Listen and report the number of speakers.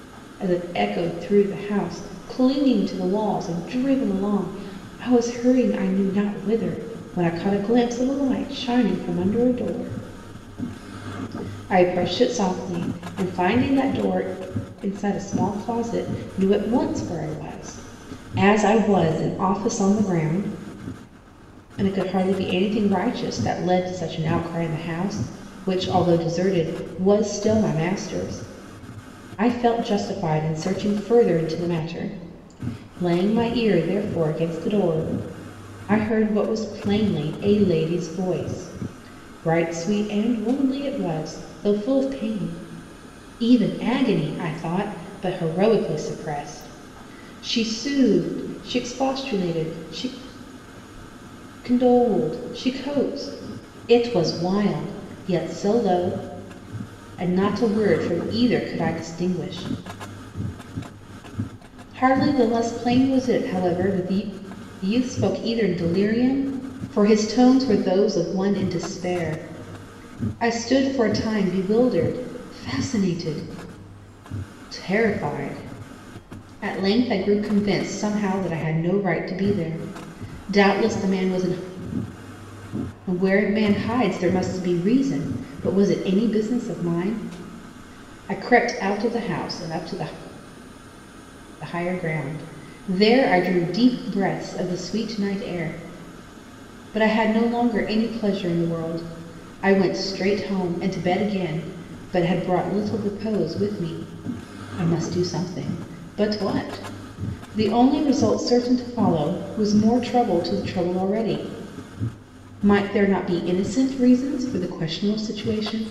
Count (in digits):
1